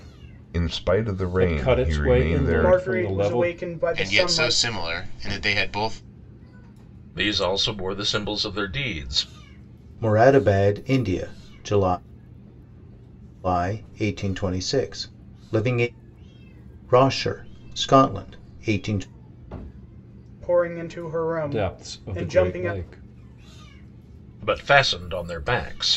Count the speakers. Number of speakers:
six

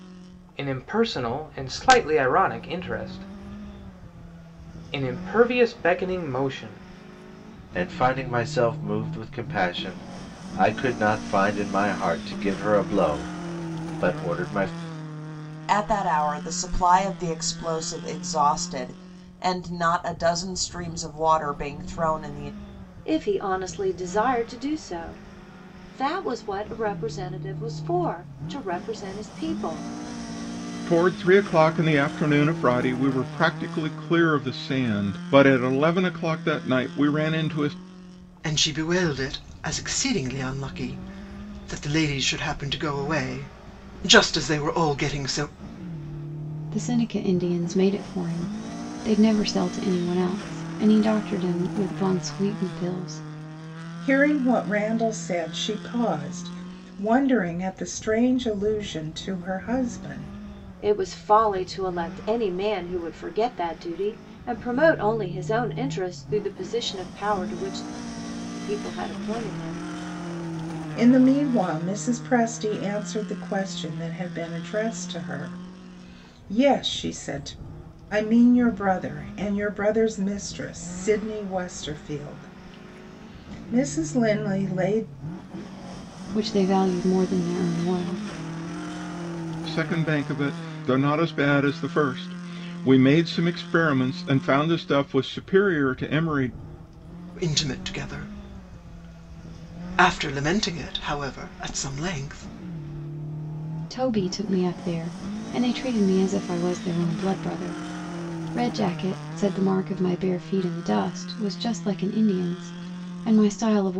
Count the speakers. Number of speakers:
eight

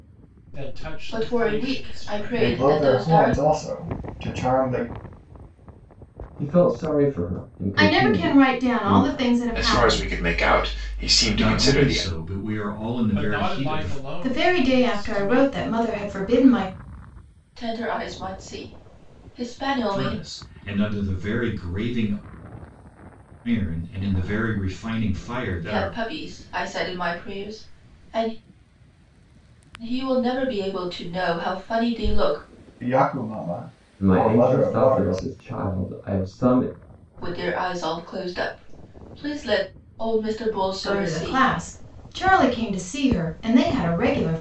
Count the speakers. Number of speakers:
seven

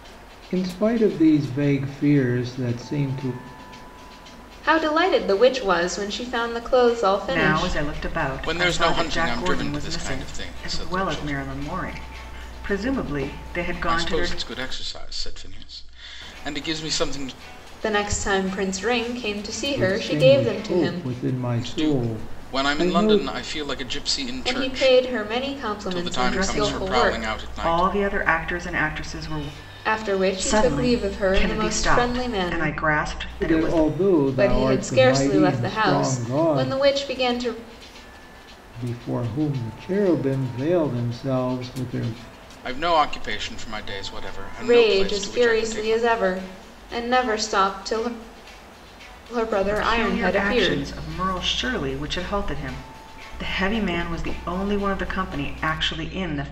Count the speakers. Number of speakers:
four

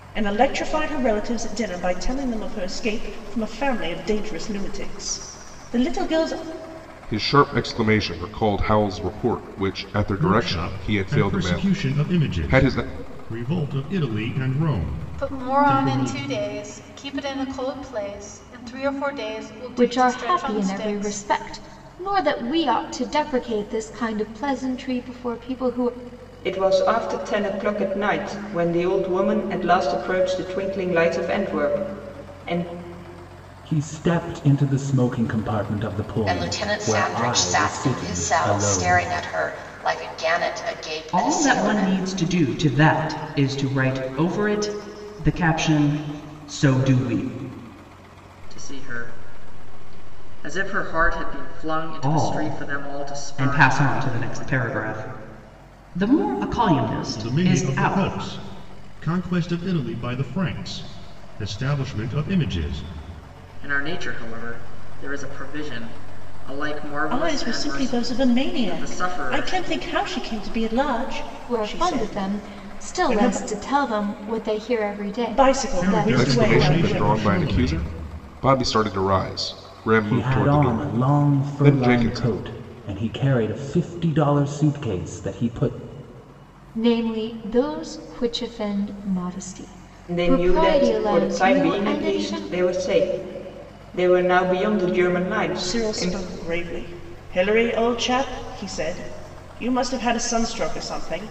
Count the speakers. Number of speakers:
ten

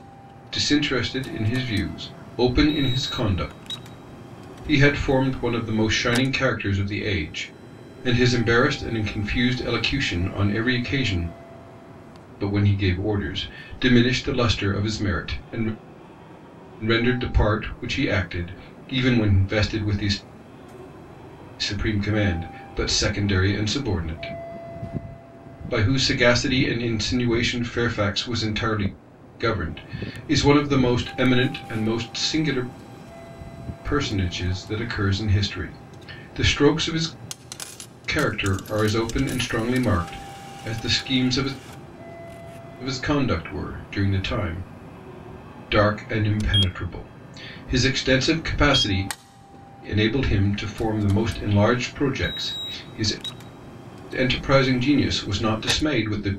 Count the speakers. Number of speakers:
one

